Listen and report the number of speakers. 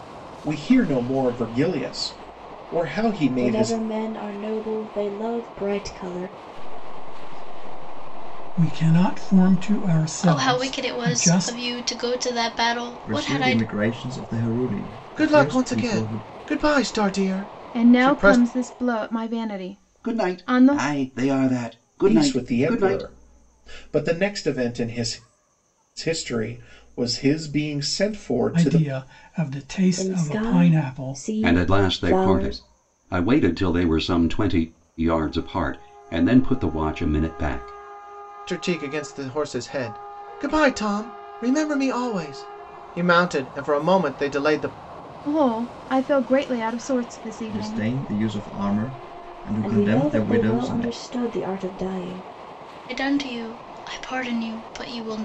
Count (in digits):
9